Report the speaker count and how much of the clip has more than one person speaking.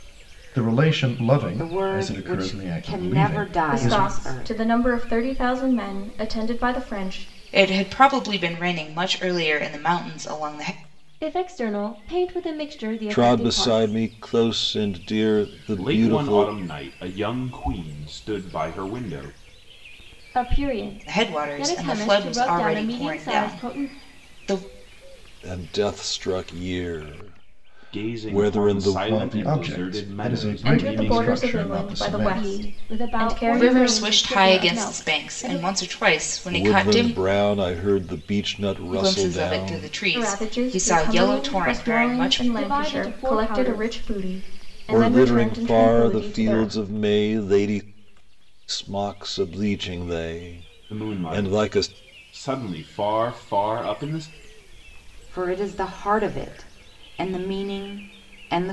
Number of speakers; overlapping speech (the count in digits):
7, about 40%